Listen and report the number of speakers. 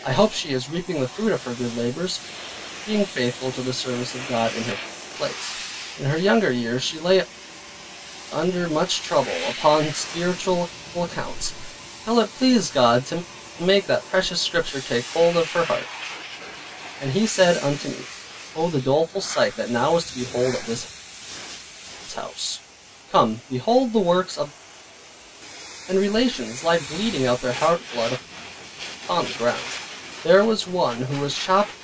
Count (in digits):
1